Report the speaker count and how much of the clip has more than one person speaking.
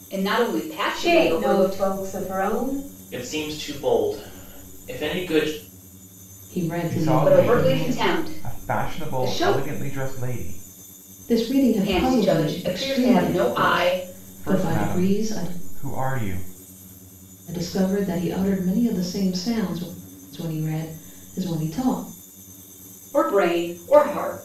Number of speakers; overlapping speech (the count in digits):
5, about 29%